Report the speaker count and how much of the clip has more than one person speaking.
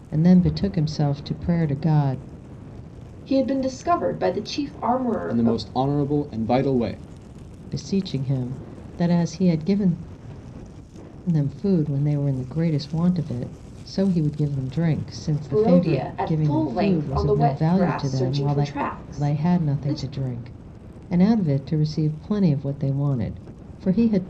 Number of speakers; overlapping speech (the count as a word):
three, about 18%